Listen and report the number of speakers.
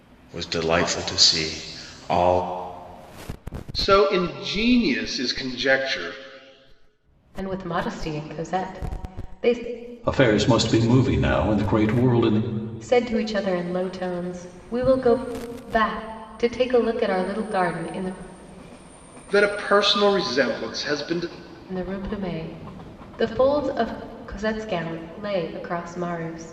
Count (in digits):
4